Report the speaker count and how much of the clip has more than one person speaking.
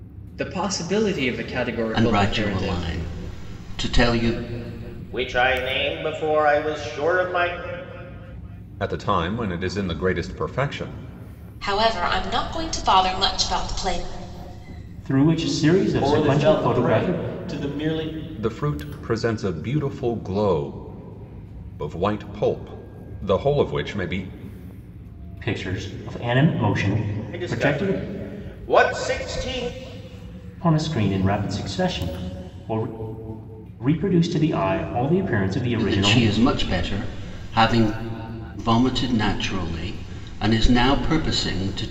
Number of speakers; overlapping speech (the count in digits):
7, about 8%